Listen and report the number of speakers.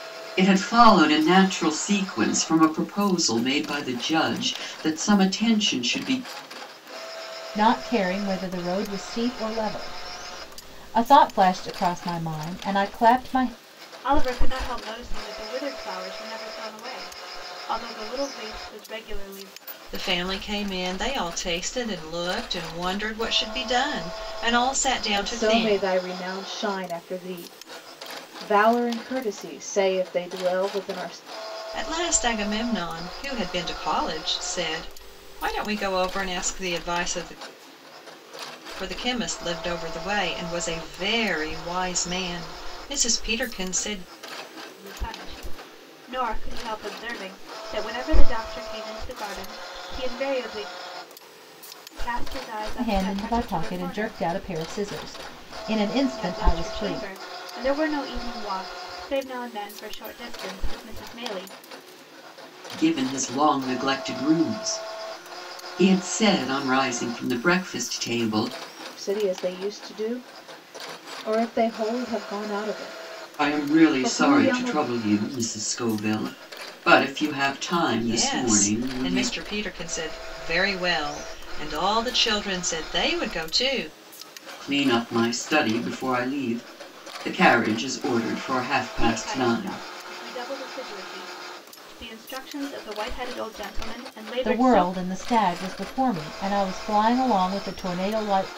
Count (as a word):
five